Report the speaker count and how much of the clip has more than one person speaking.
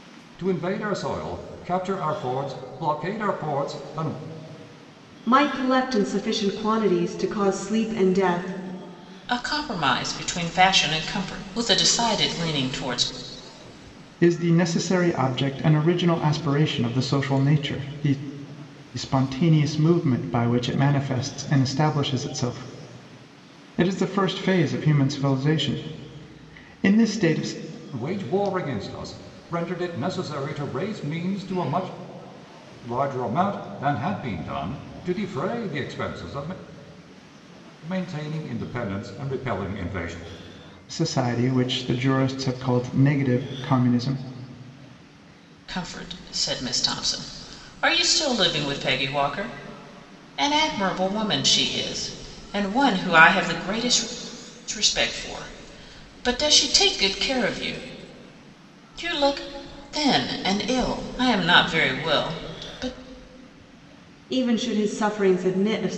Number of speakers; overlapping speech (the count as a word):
four, no overlap